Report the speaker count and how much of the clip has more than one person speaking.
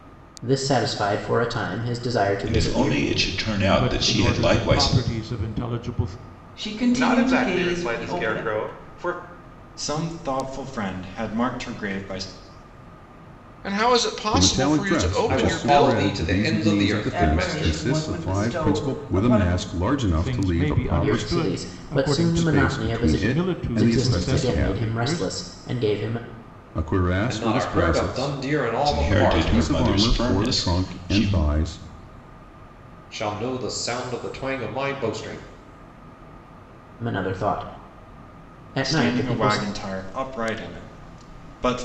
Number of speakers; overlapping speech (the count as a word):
nine, about 45%